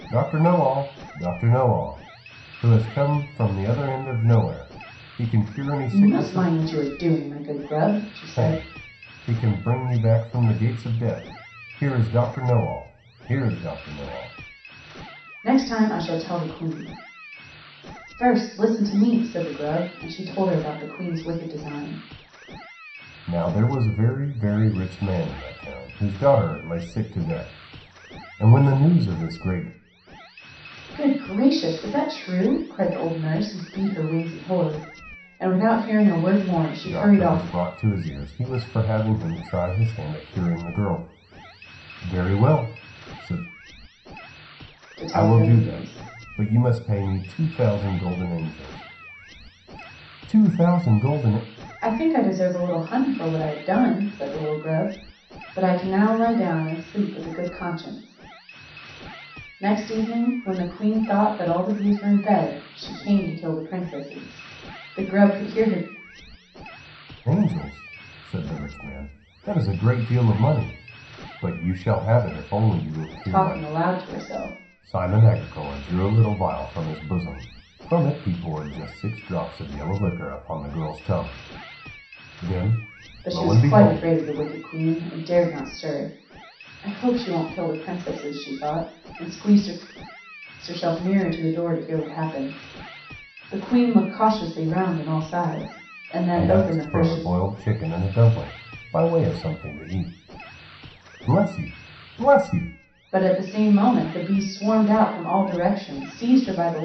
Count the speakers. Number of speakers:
two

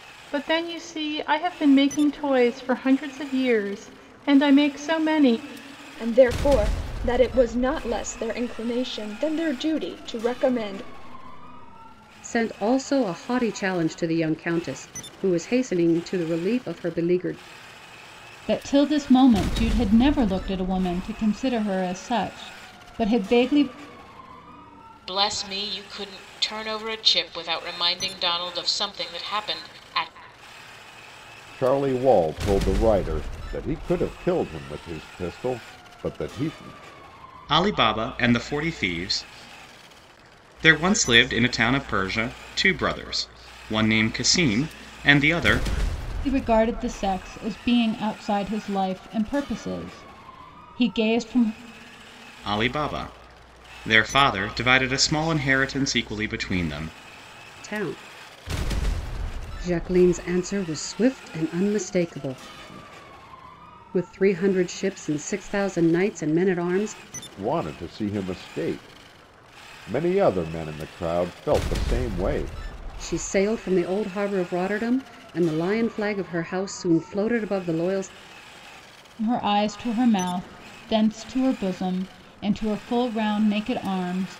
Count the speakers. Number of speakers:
seven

